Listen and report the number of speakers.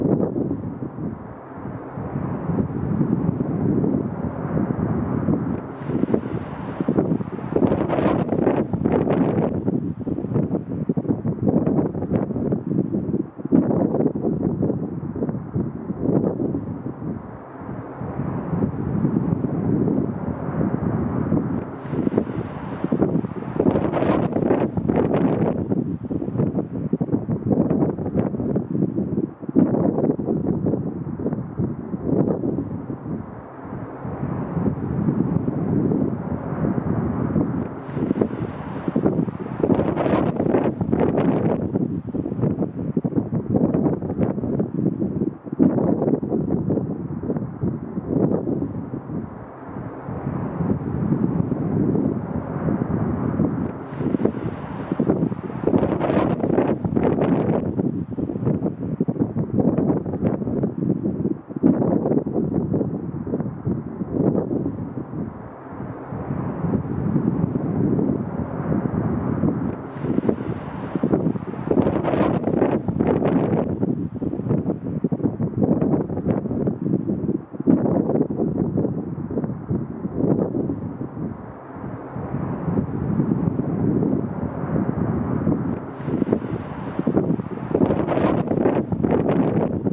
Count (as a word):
zero